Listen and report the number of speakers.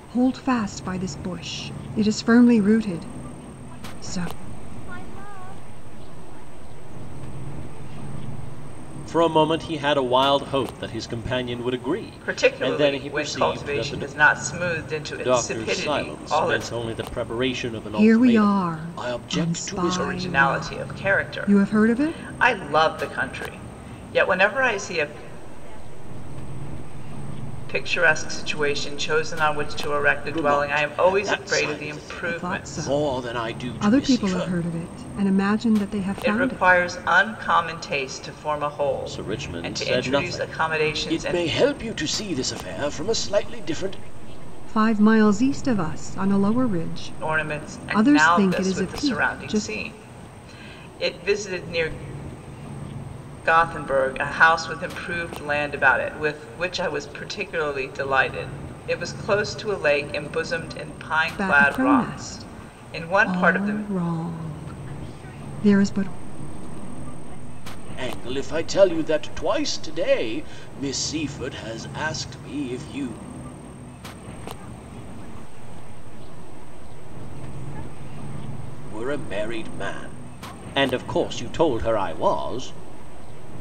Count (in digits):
4